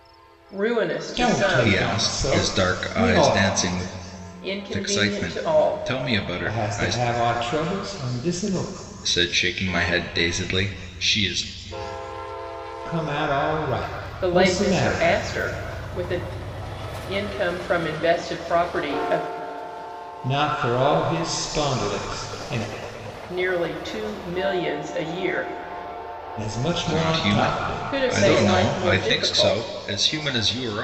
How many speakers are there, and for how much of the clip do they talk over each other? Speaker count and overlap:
three, about 25%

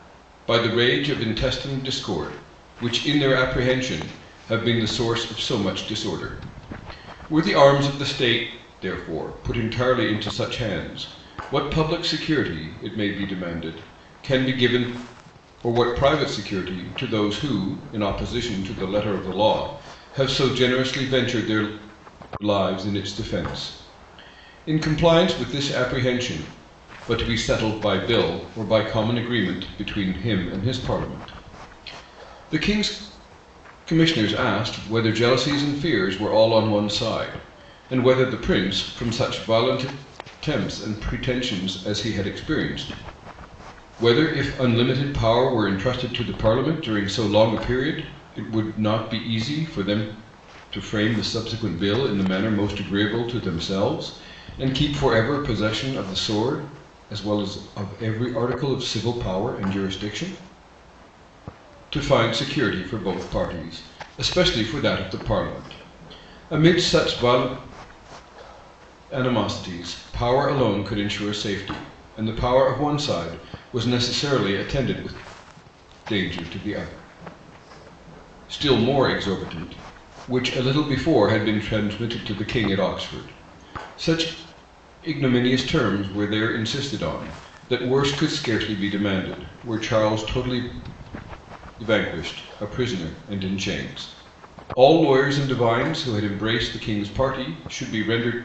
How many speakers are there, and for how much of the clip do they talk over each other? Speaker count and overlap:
one, no overlap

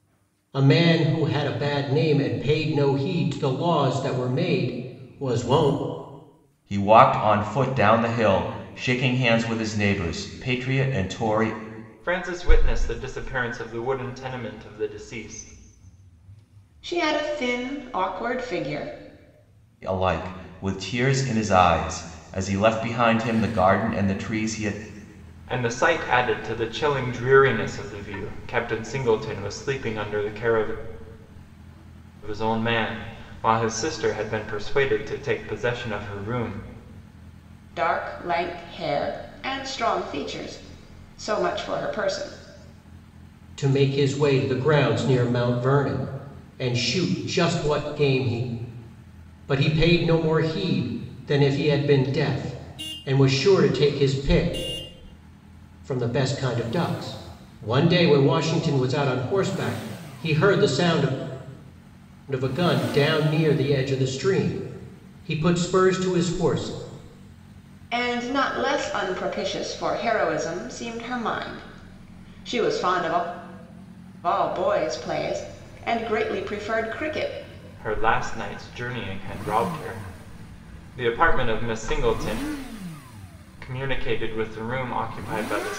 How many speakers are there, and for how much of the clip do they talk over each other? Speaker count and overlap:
four, no overlap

